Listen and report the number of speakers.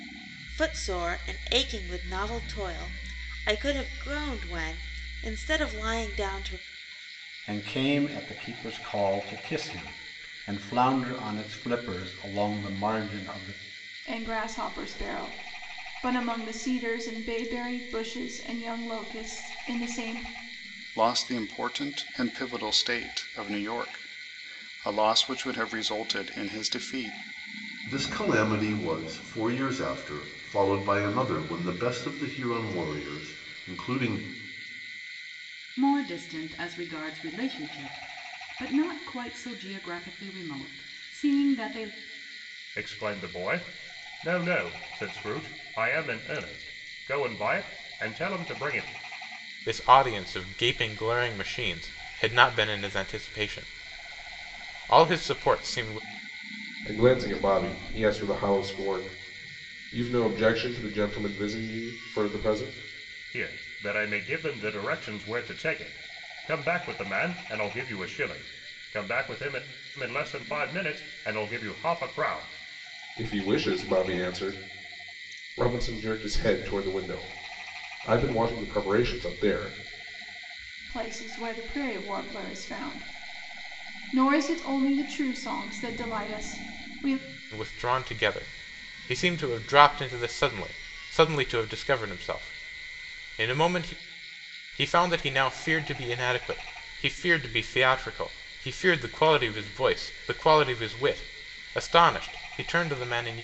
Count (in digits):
9